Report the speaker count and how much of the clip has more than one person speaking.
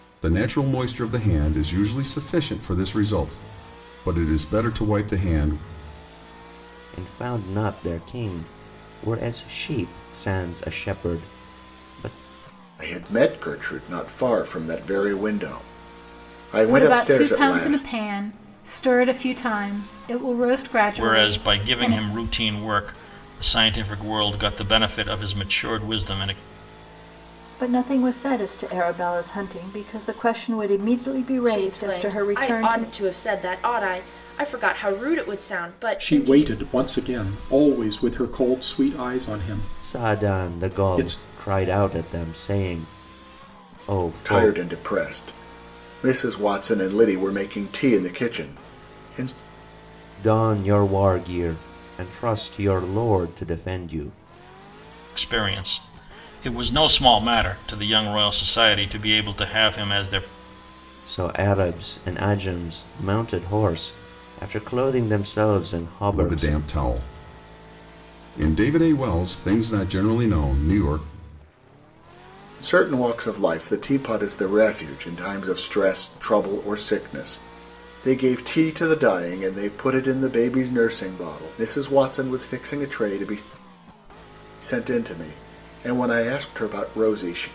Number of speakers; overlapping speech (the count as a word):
eight, about 8%